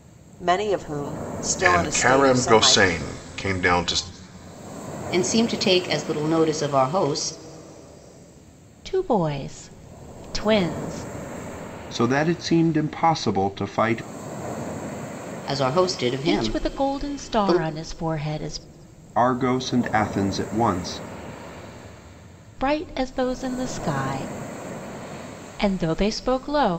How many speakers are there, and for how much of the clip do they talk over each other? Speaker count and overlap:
5, about 10%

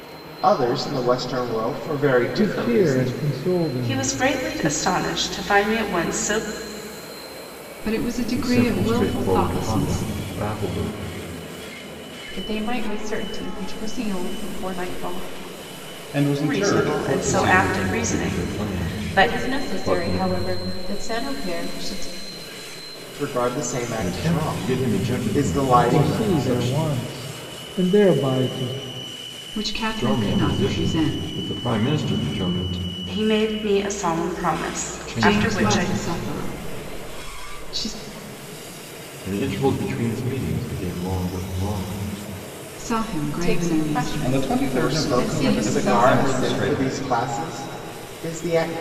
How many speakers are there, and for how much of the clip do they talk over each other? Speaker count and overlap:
7, about 34%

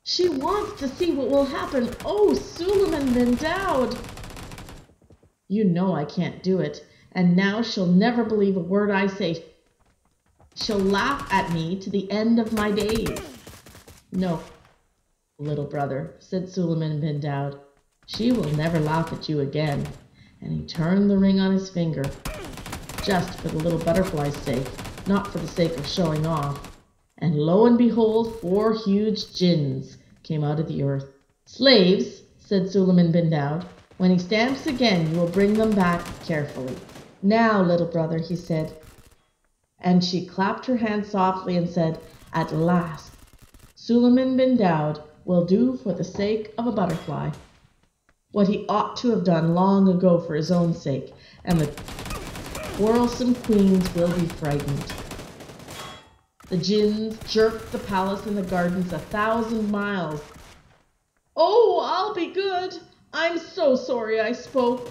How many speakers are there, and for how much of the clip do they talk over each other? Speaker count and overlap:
1, no overlap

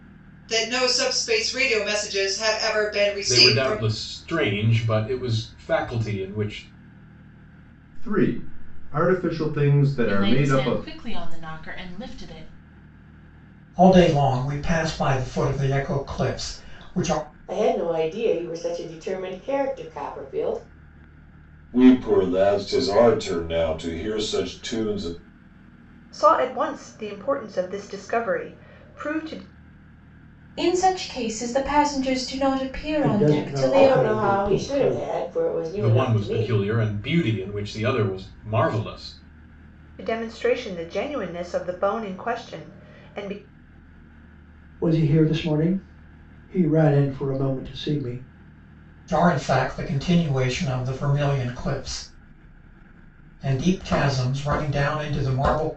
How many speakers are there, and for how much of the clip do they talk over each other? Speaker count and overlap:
10, about 8%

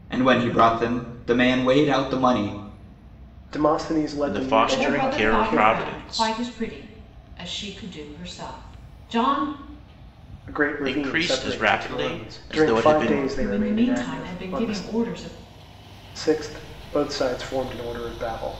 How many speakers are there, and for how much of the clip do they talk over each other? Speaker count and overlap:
4, about 33%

